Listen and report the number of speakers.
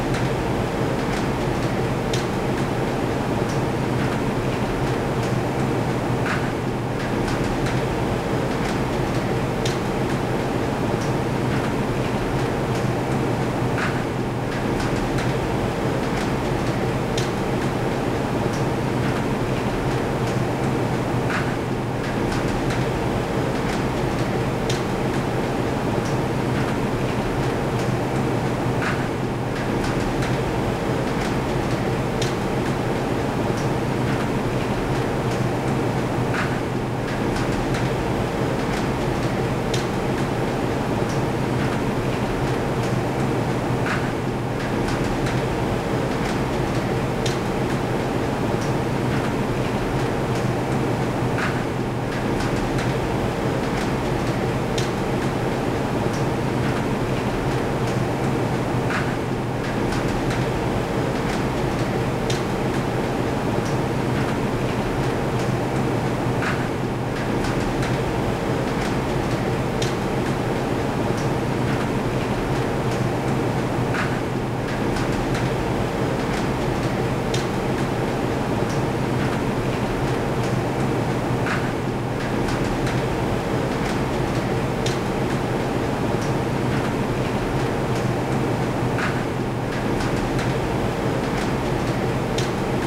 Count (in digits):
0